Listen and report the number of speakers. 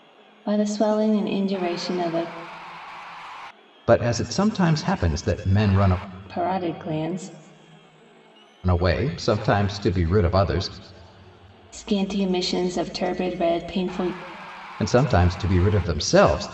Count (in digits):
2